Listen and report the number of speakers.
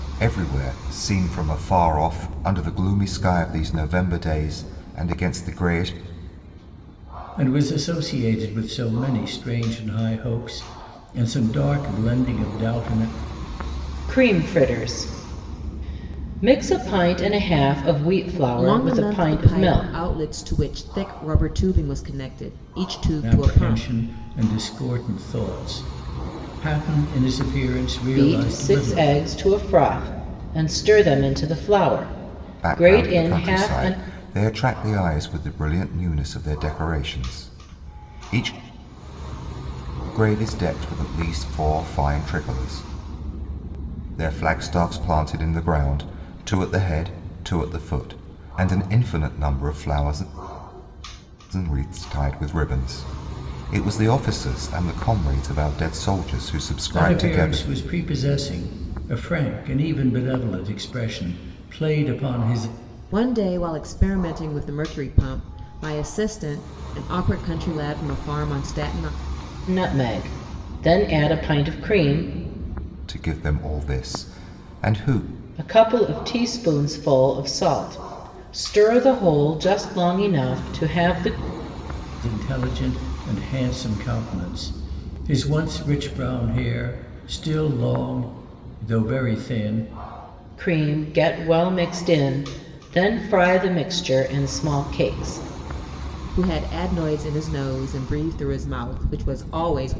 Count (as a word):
four